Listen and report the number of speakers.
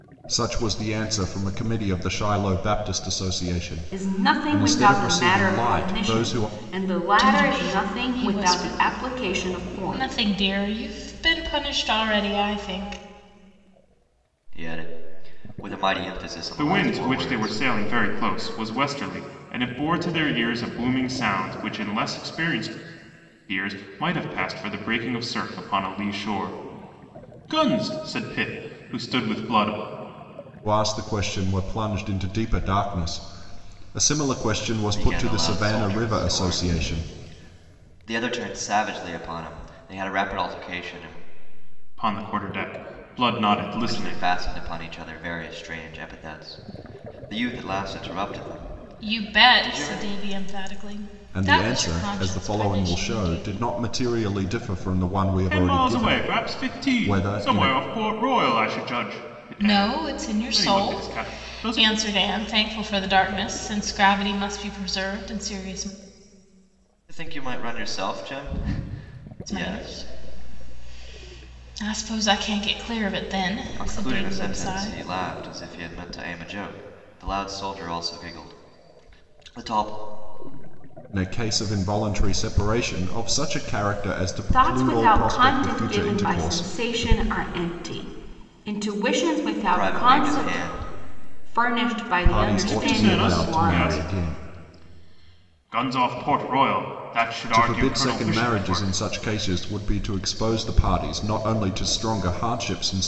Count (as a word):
five